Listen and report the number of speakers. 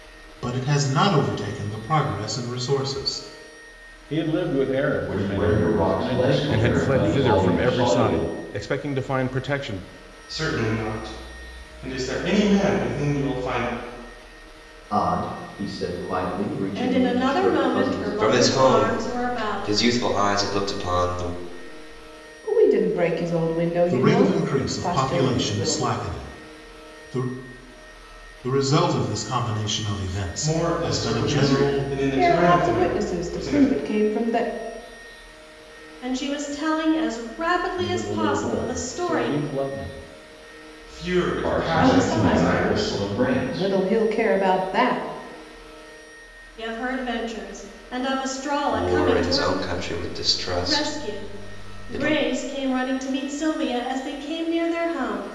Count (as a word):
nine